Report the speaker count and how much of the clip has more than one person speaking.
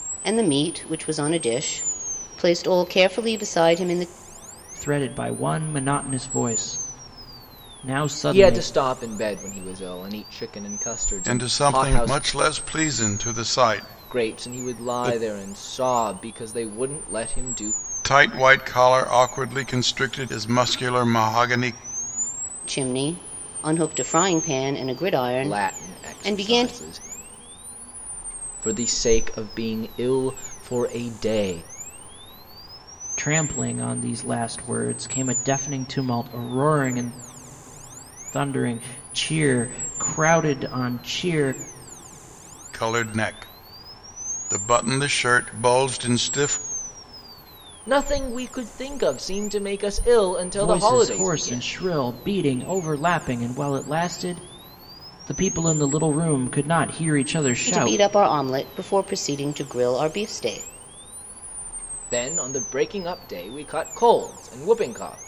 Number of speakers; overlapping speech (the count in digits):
4, about 9%